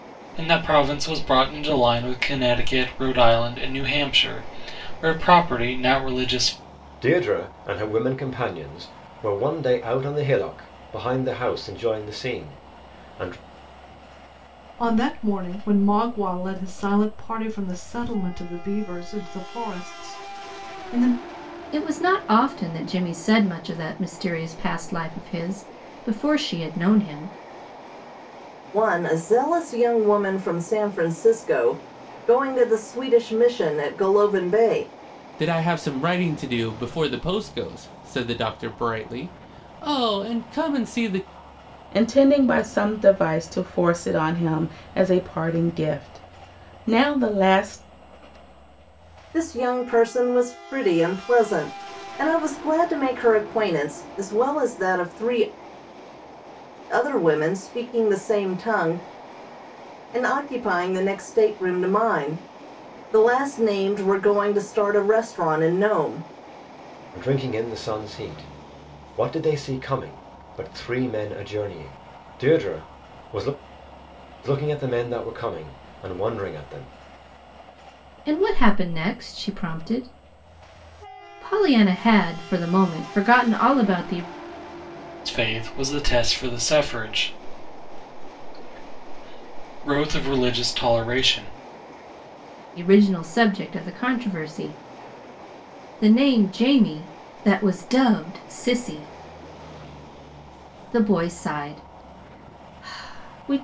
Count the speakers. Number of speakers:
7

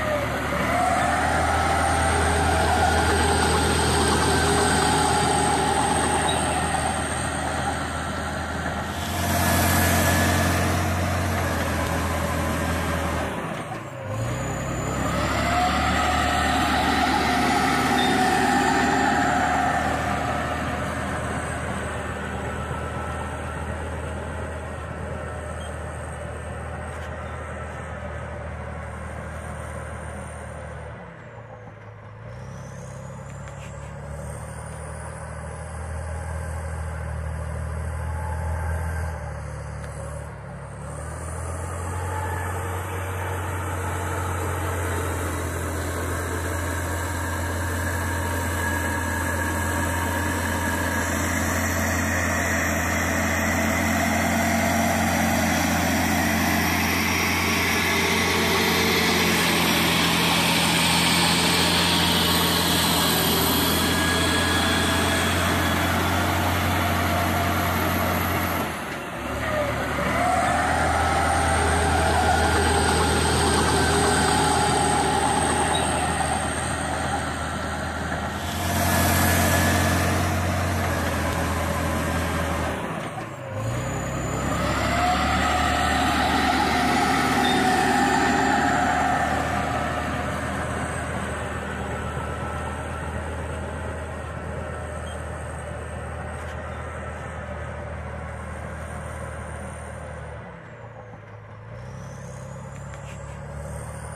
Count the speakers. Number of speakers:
0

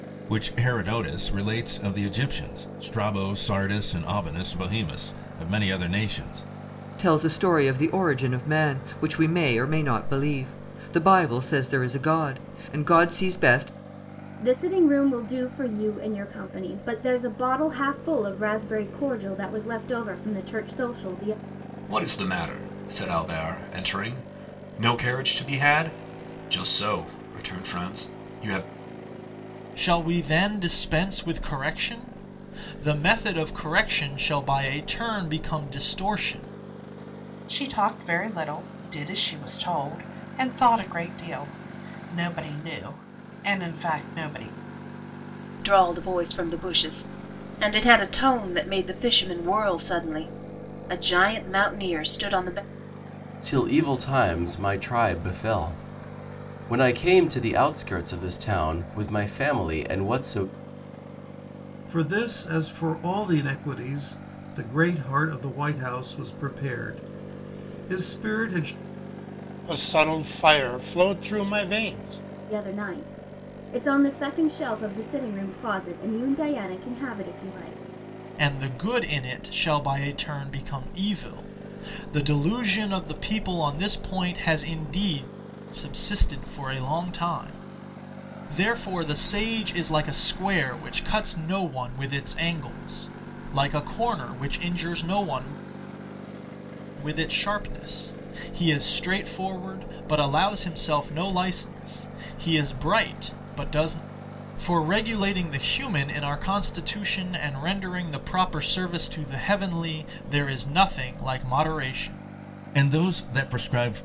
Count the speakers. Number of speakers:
10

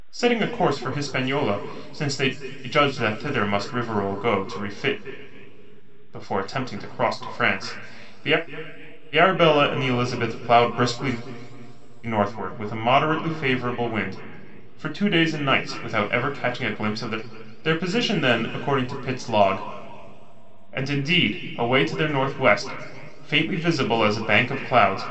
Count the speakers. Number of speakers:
1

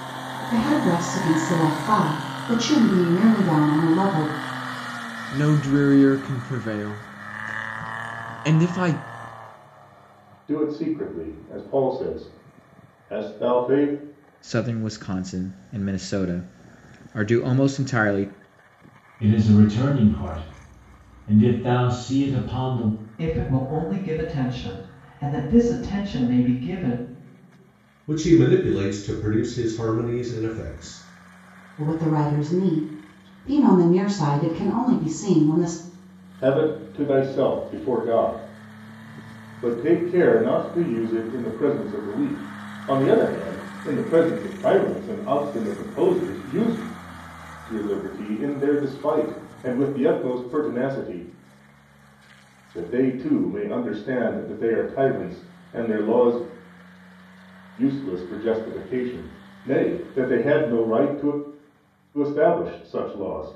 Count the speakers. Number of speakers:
7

